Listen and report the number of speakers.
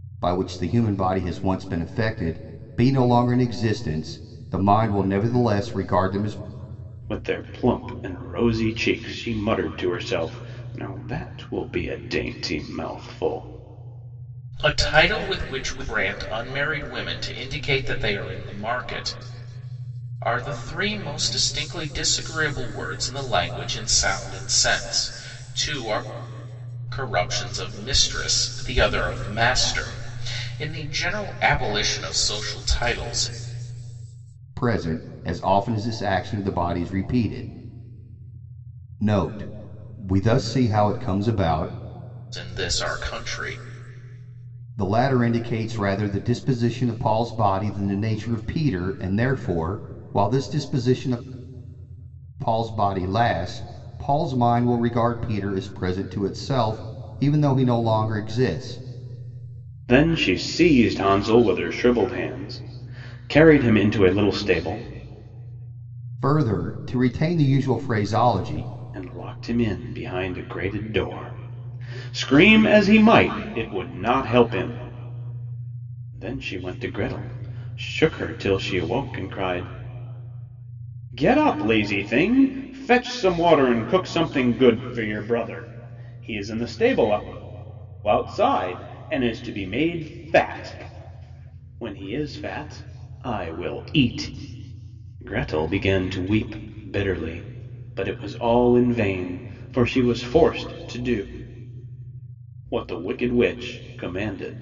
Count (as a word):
three